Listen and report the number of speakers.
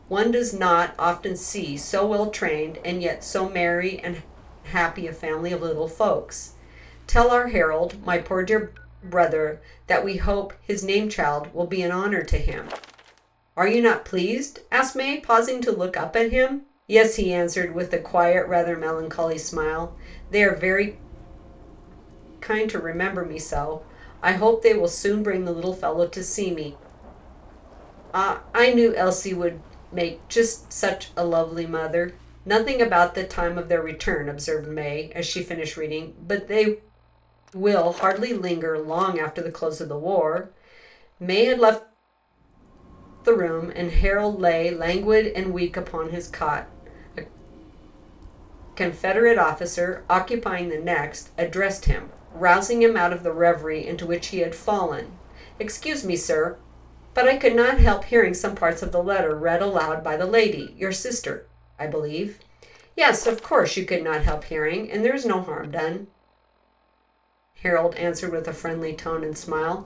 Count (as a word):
one